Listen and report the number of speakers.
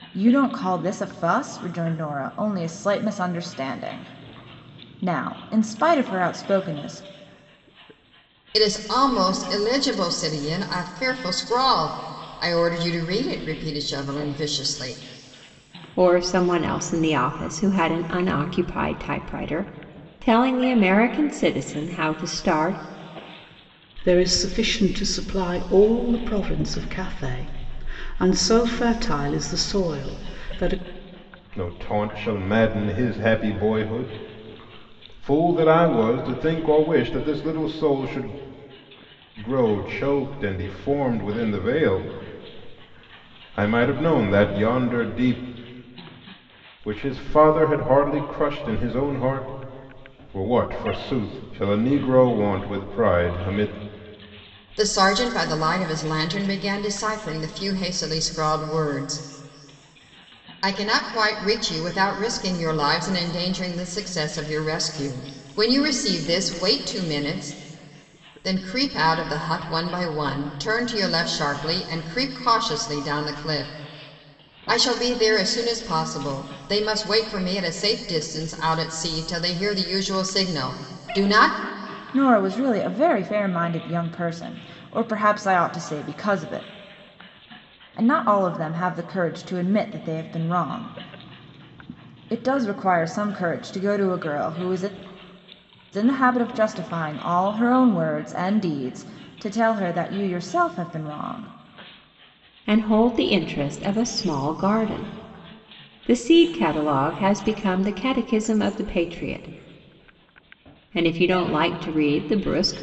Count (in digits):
5